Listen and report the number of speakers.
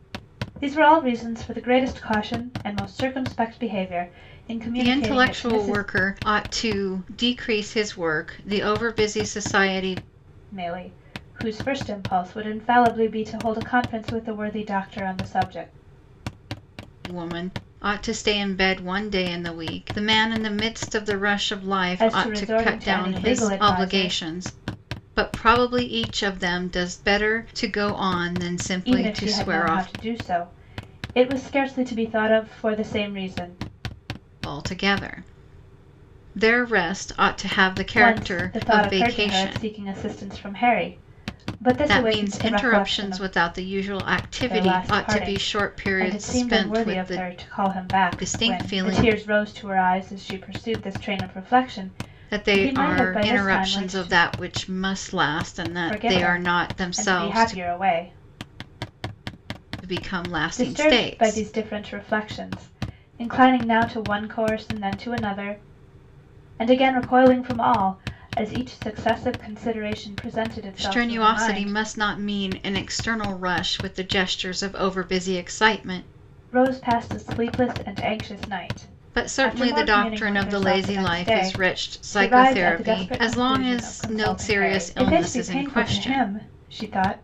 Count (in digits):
2